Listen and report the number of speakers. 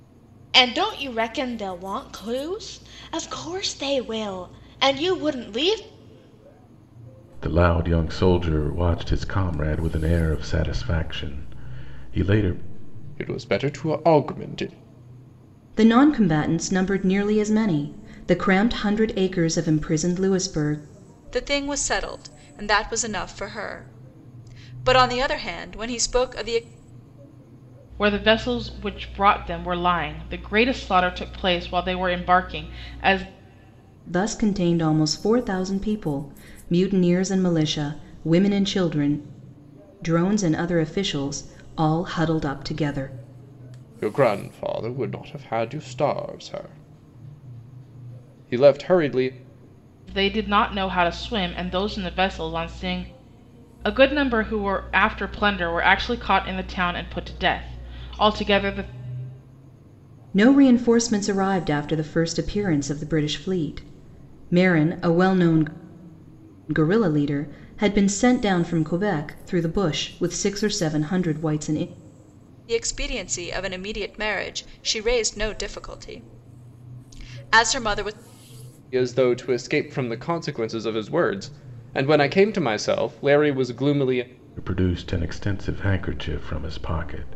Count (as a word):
six